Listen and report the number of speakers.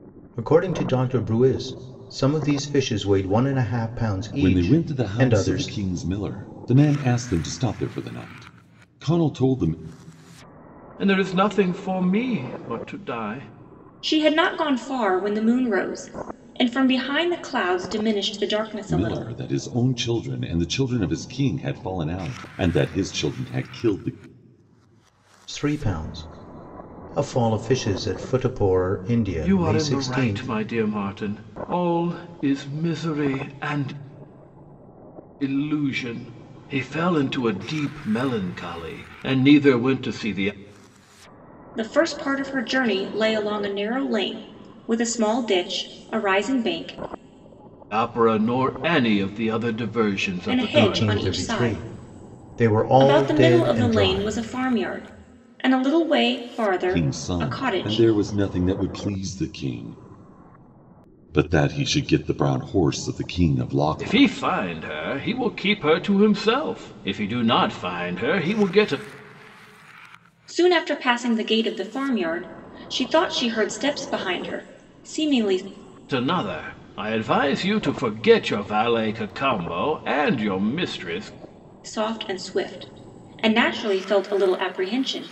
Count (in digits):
4